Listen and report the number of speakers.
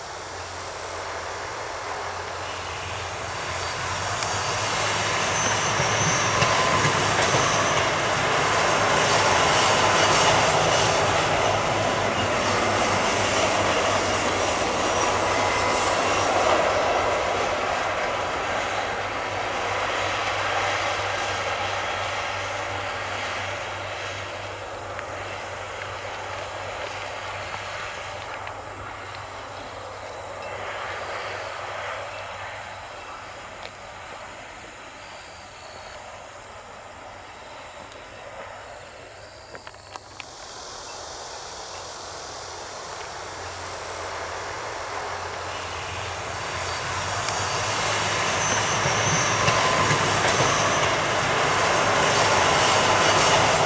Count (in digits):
0